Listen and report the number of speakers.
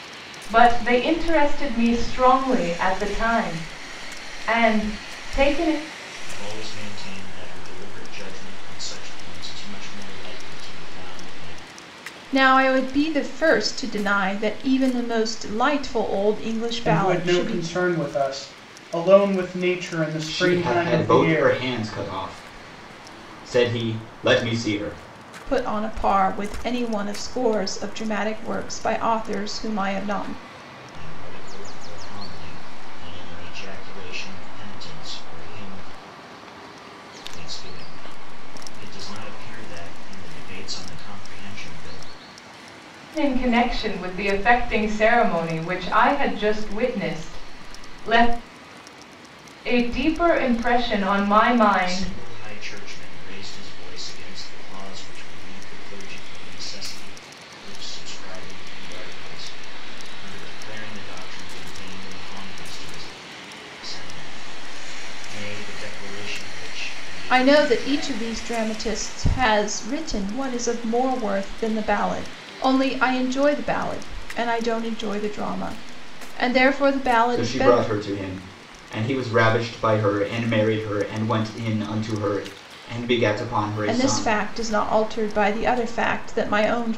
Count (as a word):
five